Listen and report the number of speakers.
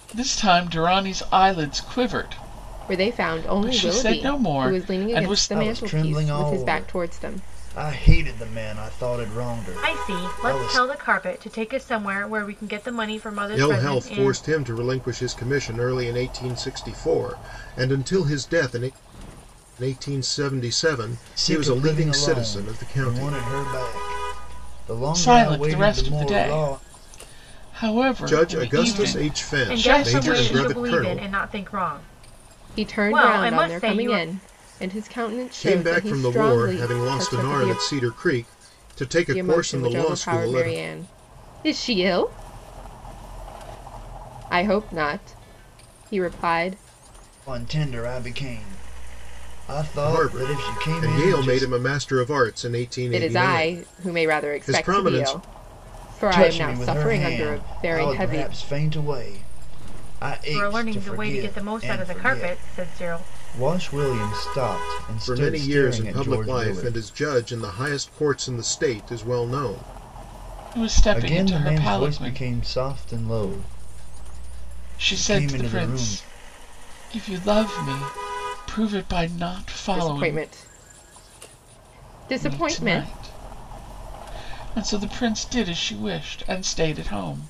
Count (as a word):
five